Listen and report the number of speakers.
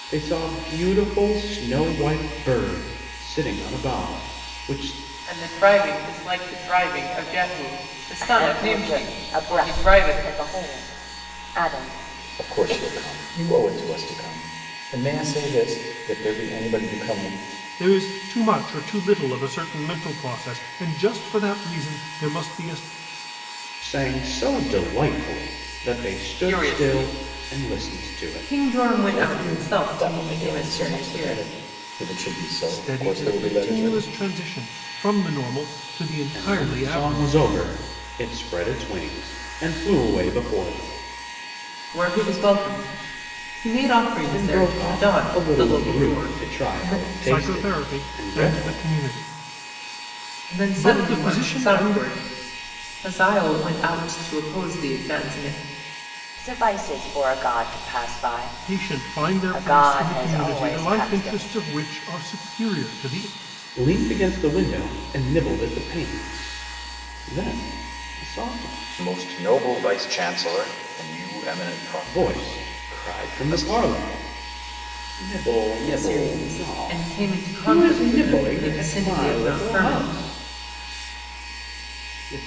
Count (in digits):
5